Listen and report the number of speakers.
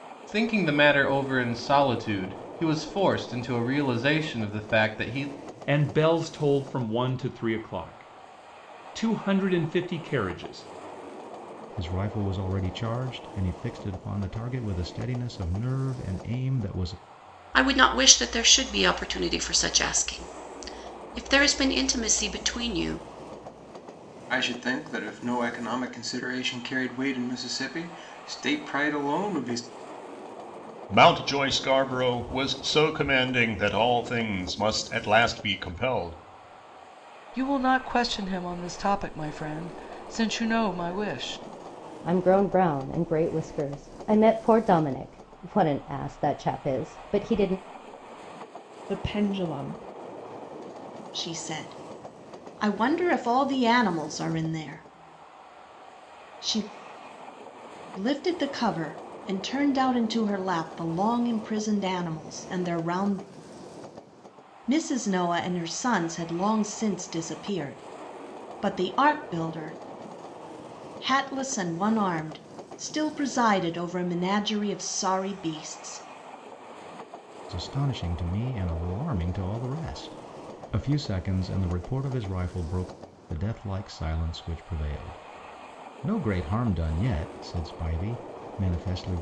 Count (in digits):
10